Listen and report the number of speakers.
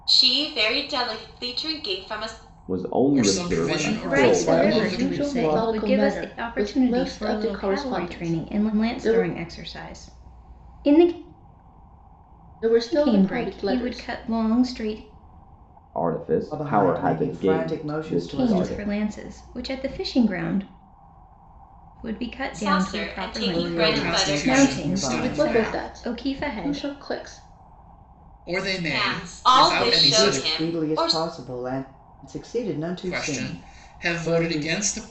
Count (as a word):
six